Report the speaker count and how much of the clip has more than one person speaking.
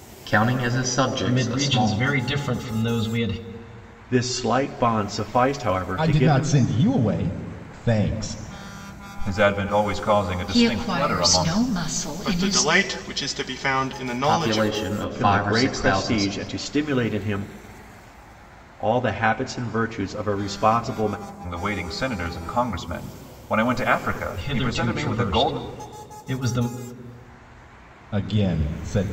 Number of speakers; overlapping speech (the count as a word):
seven, about 20%